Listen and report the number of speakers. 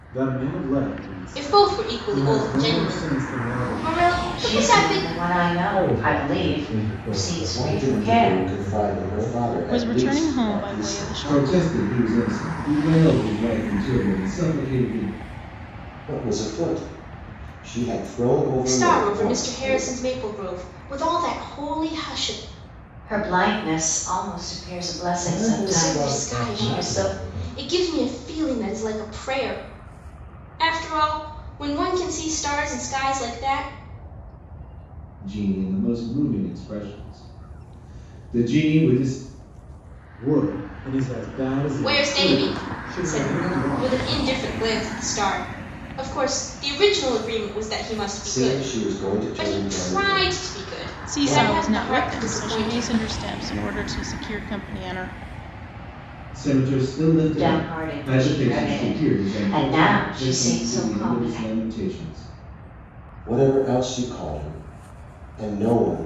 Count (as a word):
seven